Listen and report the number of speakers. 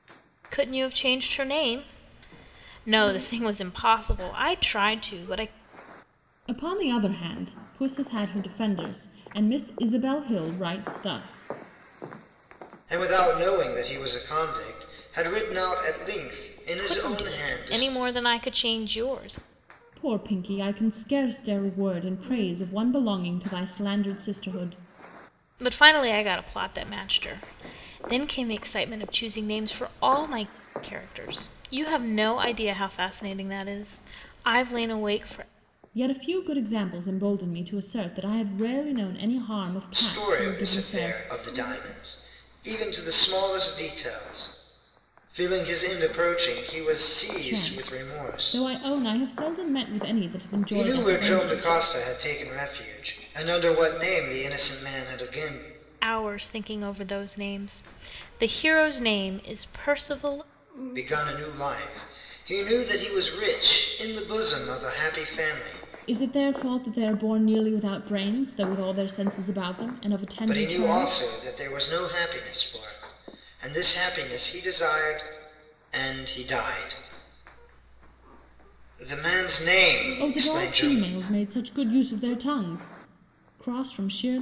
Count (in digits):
3